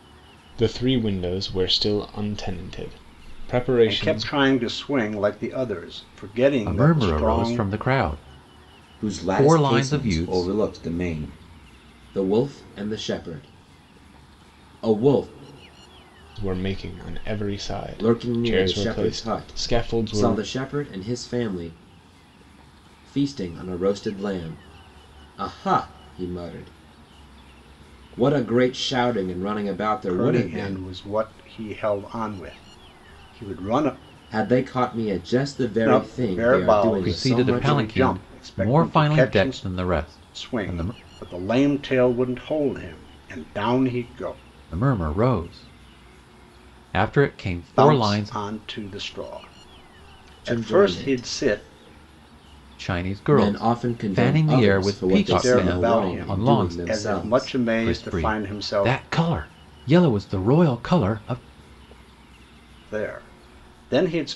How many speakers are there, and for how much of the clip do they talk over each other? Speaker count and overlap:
4, about 29%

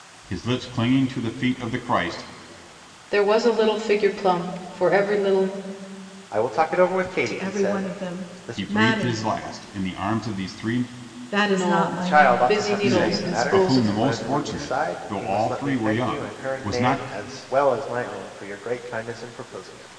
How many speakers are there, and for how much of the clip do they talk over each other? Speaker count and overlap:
4, about 37%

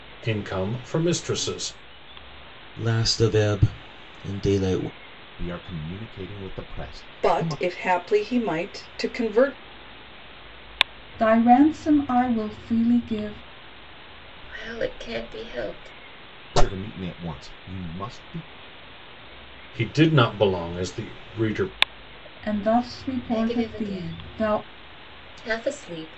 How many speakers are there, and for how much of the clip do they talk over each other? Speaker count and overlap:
6, about 8%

